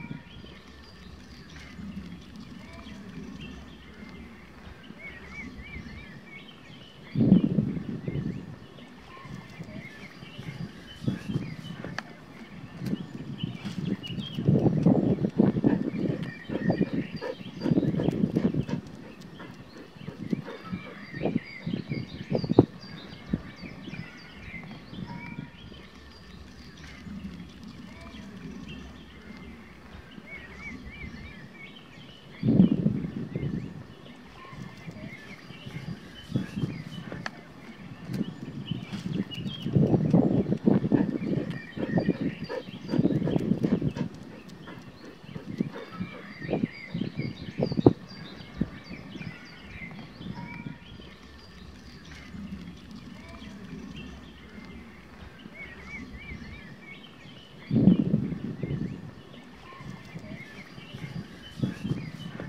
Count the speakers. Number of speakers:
0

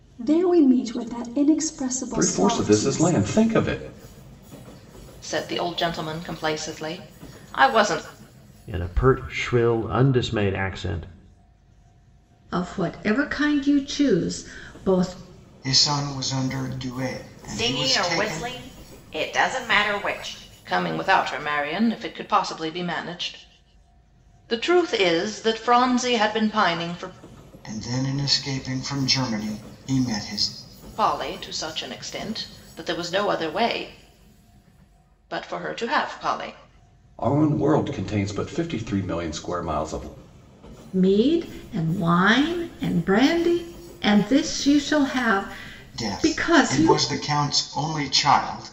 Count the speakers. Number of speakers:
7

